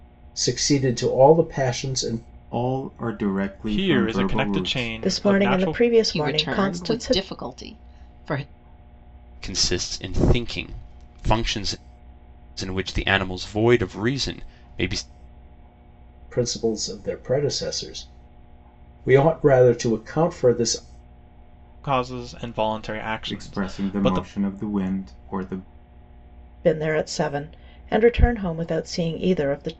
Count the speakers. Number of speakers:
six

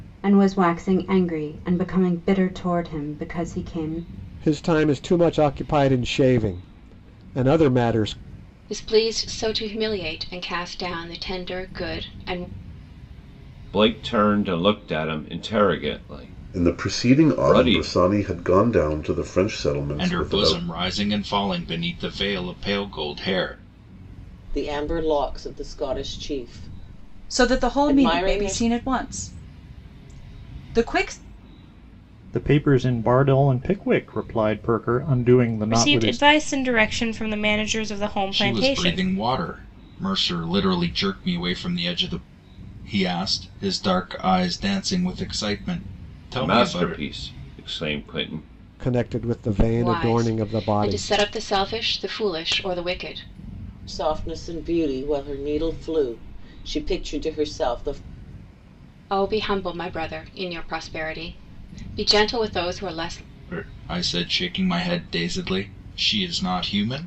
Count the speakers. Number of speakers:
ten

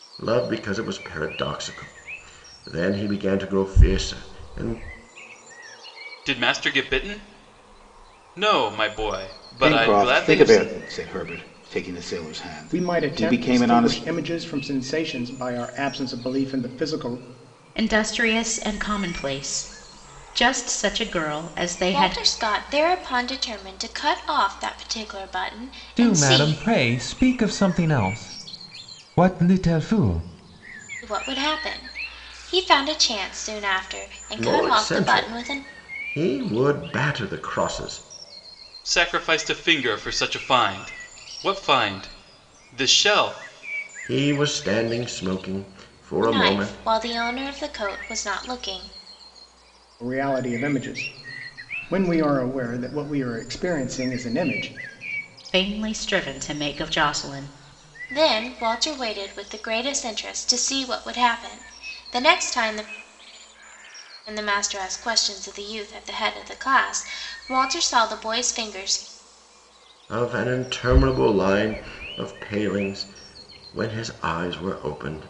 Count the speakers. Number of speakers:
seven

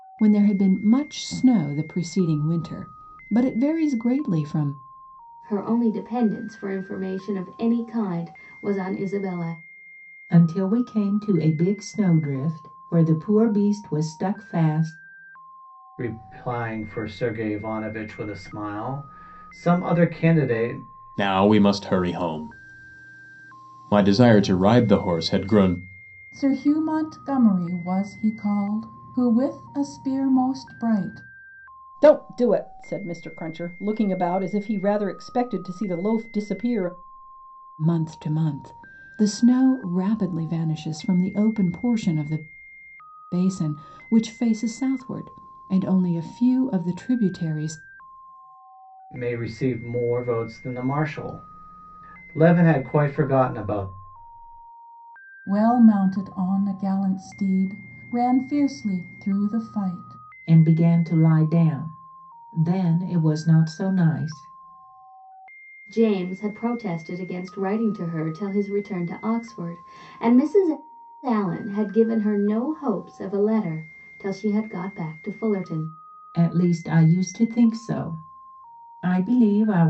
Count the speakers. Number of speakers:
seven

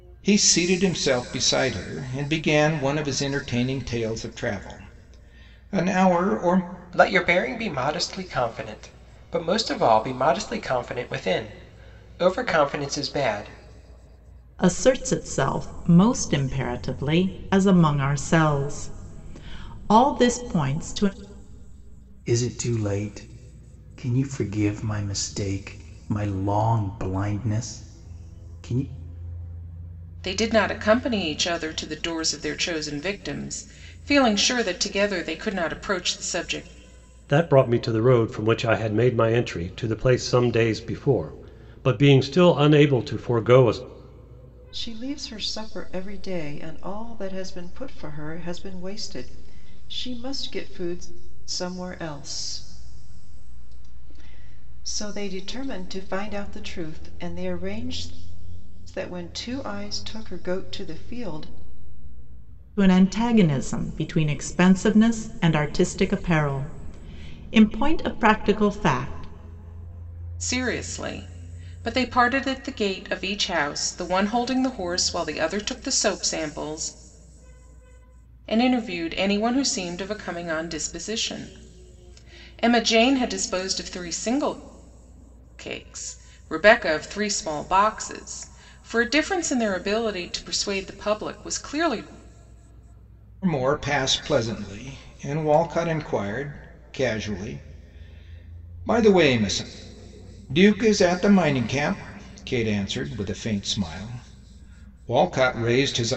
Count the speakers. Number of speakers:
seven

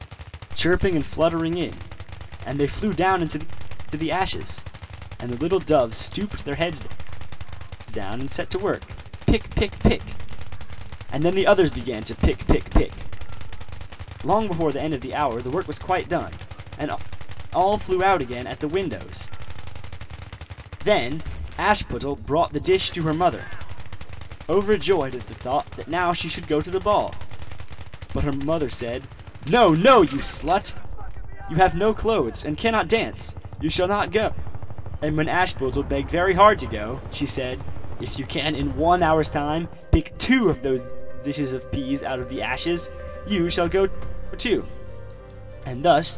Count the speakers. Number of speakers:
one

